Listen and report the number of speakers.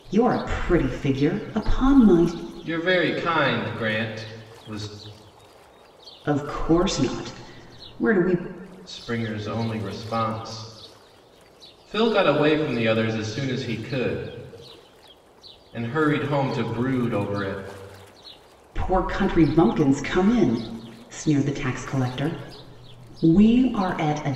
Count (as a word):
two